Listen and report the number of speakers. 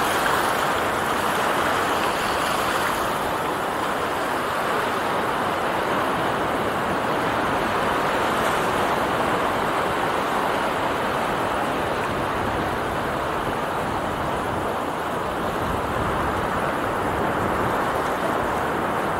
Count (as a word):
zero